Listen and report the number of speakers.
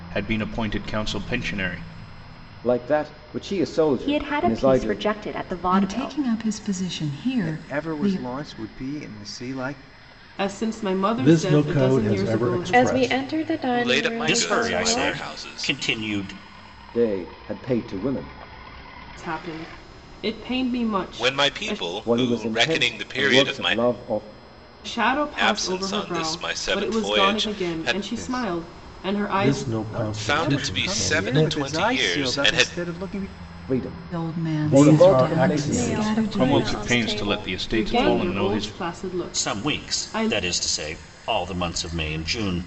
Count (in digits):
10